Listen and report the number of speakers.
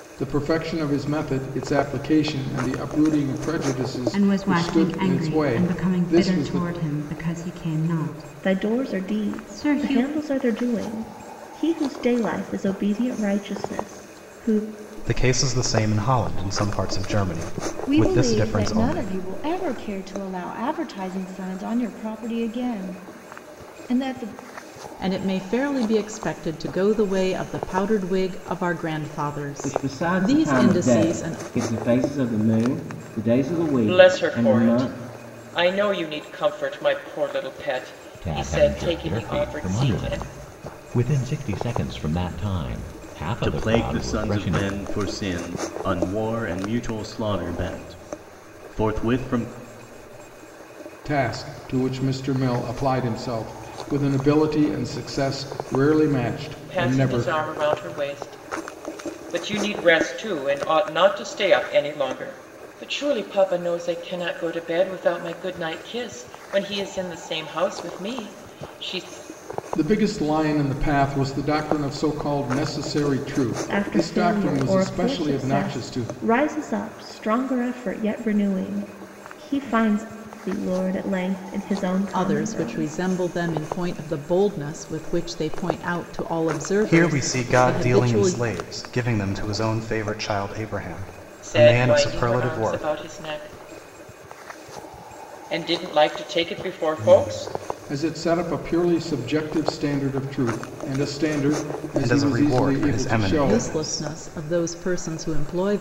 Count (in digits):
10